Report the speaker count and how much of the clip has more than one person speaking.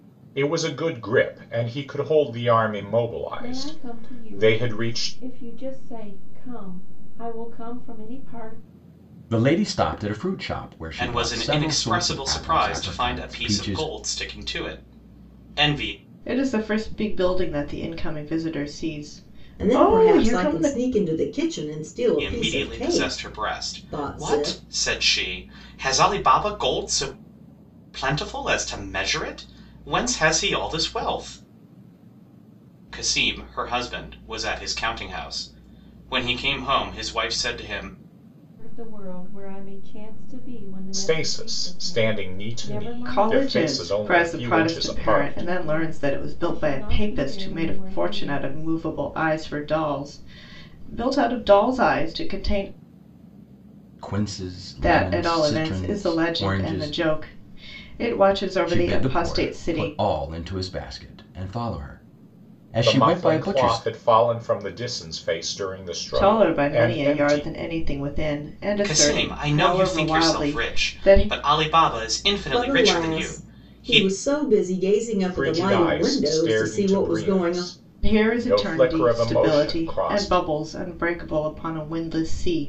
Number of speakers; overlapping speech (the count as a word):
six, about 38%